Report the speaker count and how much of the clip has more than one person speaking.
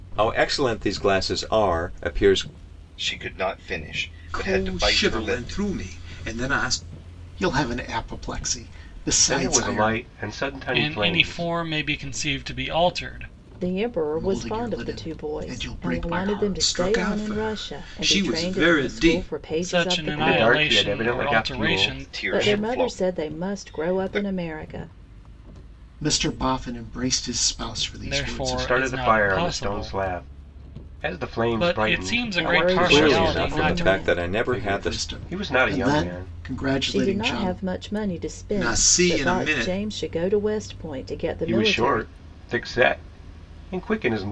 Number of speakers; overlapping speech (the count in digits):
7, about 50%